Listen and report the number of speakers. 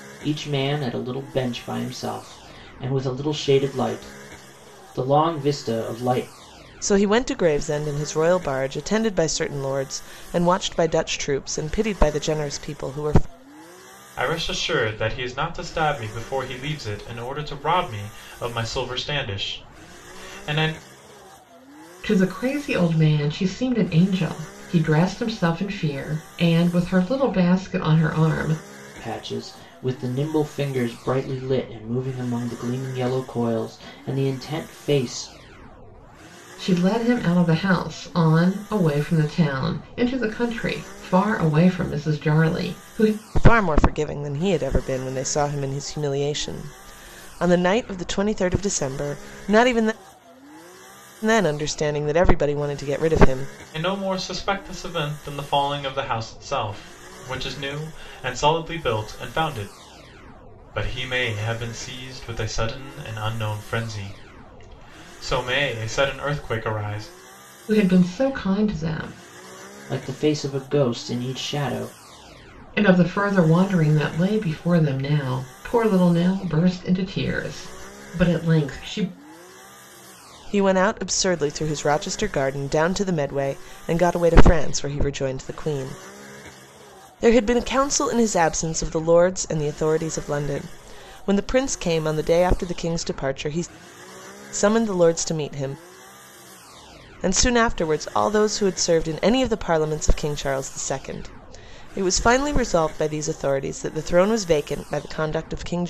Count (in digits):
4